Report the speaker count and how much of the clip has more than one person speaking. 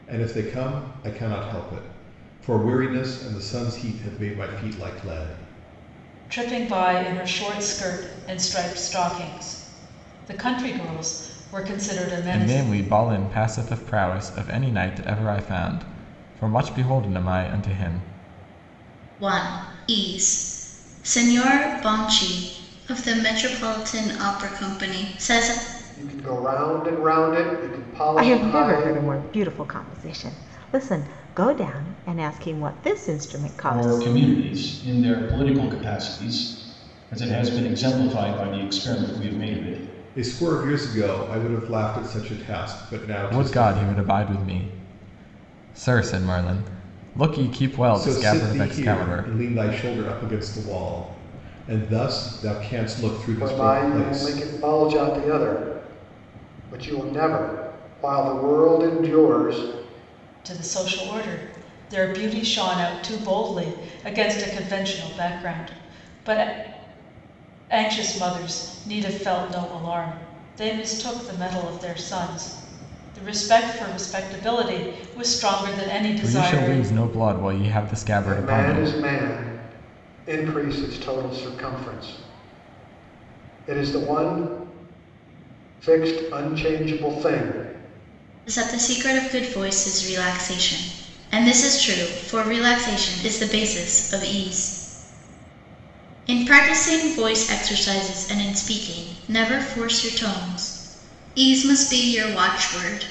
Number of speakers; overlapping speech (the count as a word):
seven, about 6%